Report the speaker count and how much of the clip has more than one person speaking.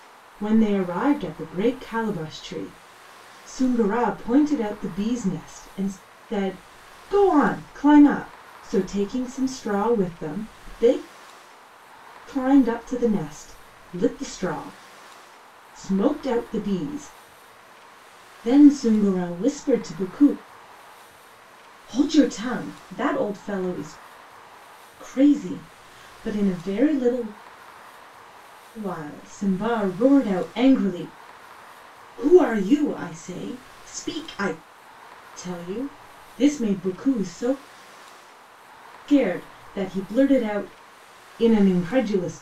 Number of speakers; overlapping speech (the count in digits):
1, no overlap